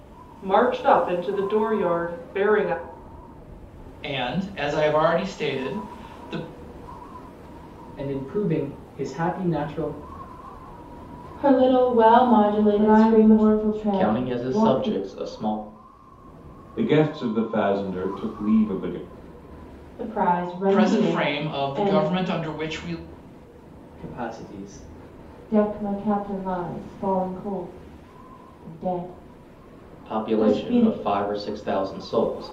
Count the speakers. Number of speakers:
7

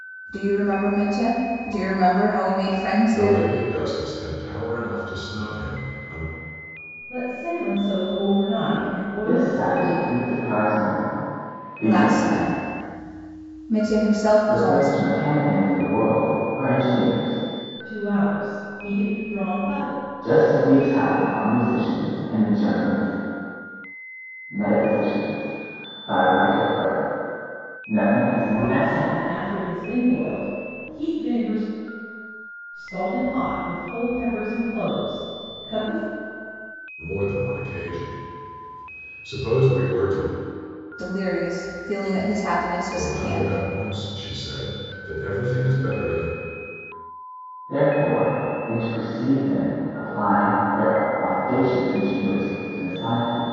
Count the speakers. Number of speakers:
4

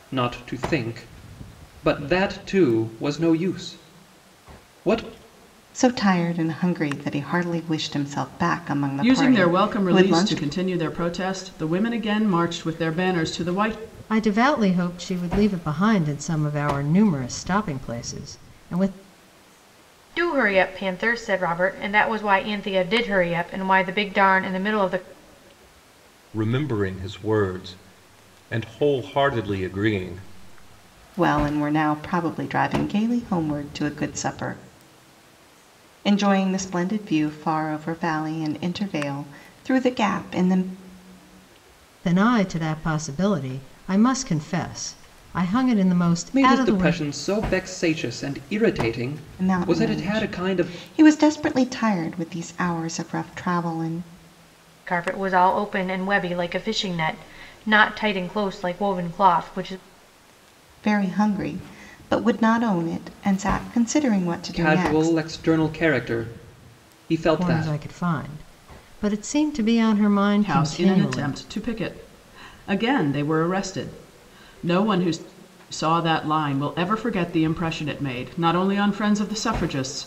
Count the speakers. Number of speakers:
6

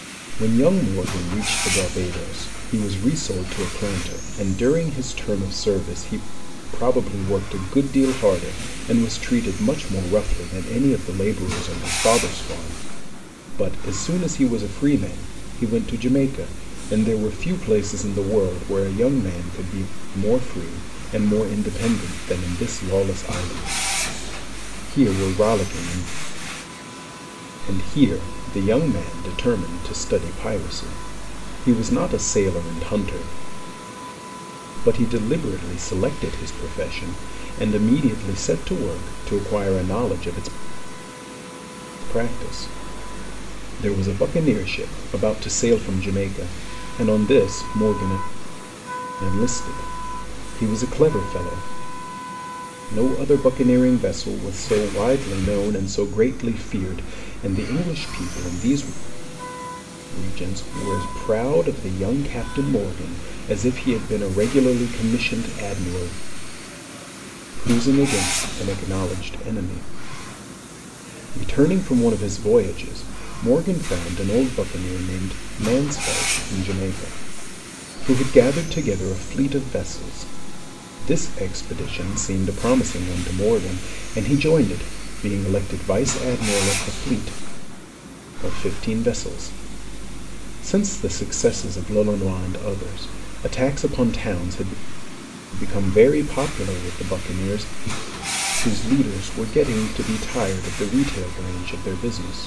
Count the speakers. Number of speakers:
1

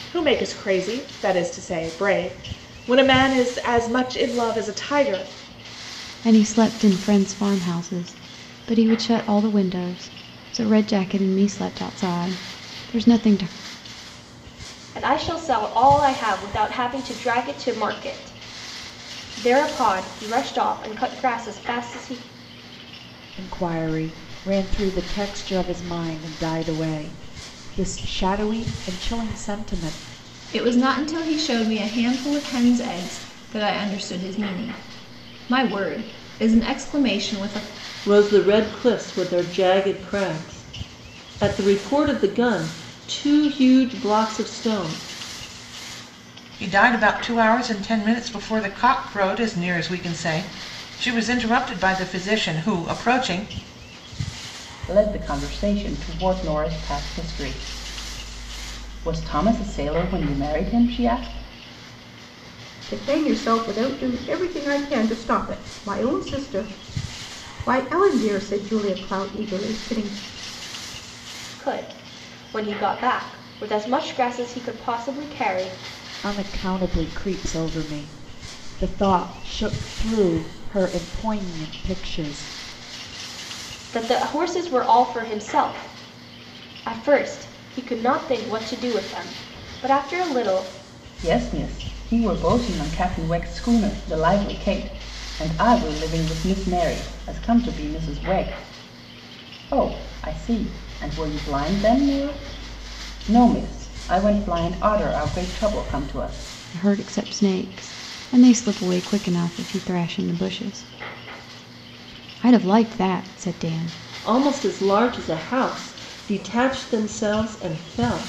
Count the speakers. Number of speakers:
9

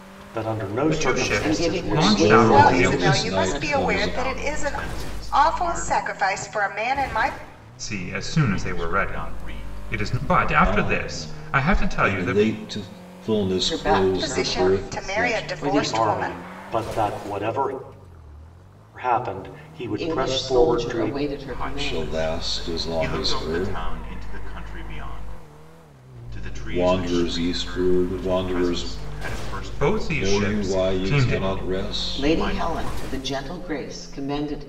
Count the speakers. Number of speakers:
6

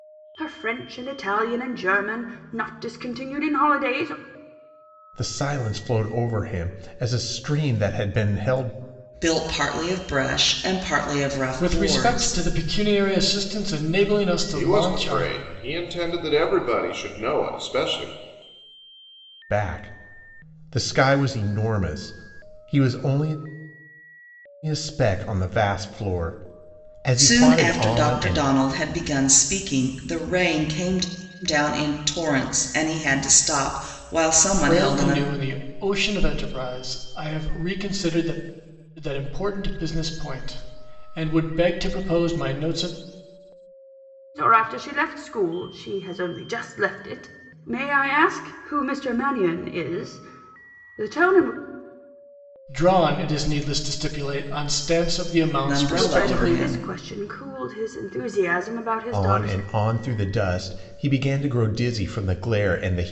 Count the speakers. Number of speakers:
5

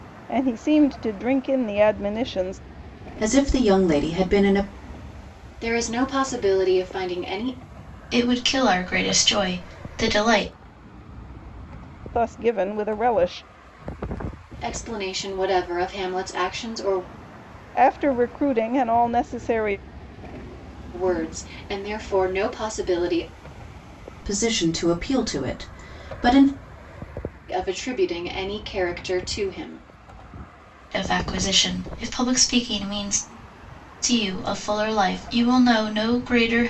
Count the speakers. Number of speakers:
4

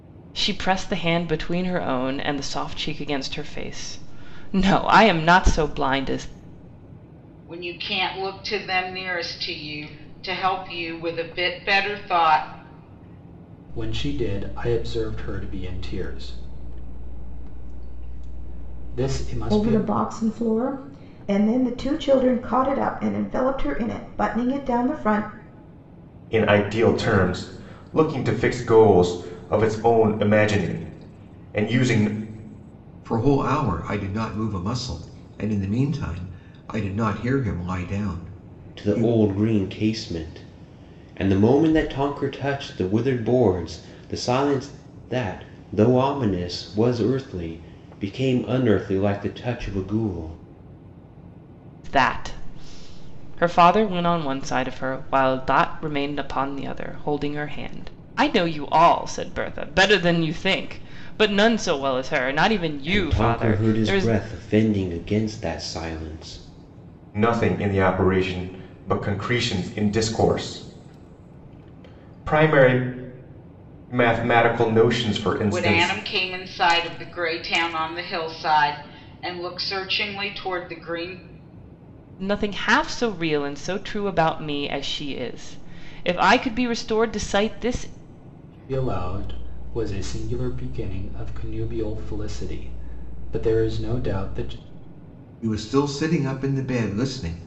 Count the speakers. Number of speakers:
7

